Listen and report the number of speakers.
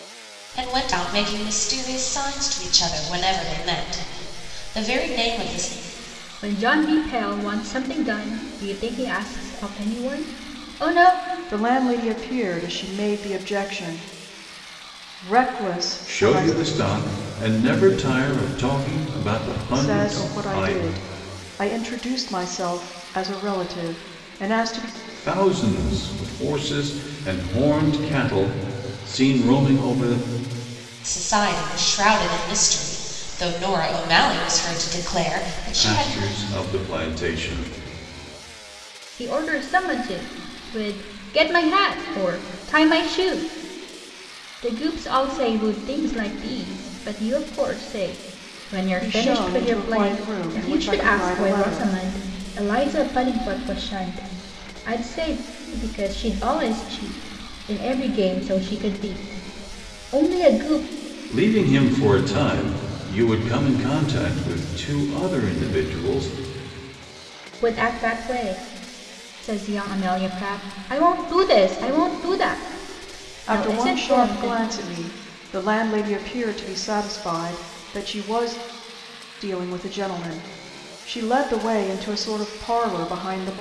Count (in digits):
4